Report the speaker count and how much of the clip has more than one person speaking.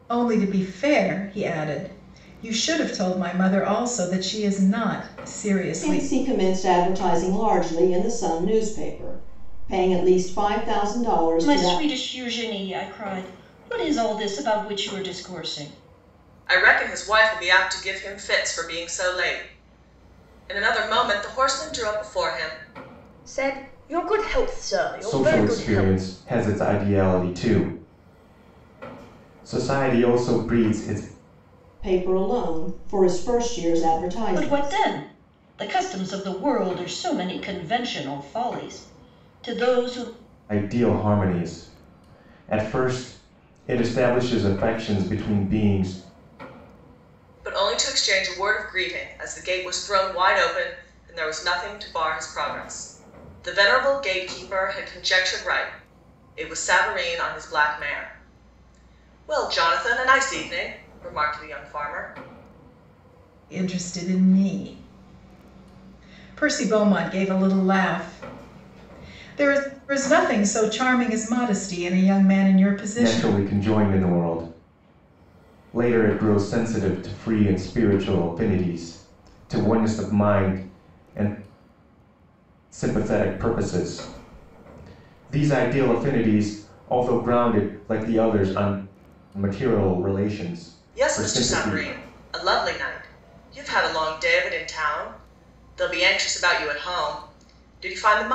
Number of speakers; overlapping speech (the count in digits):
6, about 4%